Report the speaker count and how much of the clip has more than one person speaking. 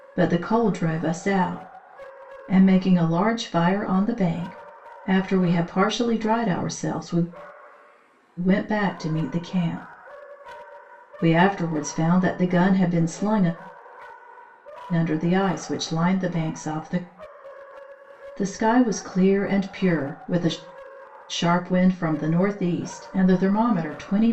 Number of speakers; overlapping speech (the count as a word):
one, no overlap